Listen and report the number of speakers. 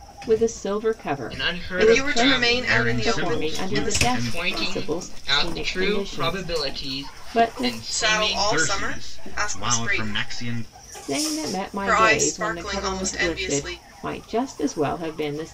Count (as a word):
four